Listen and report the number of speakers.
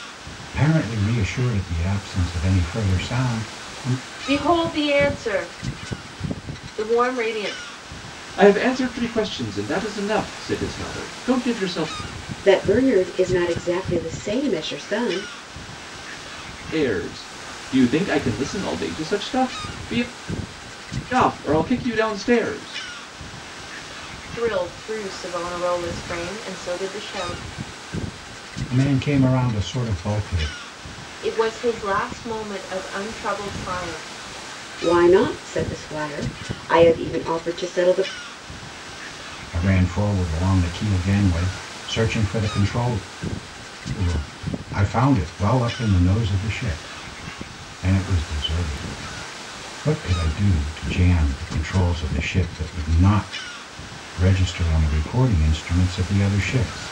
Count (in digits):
4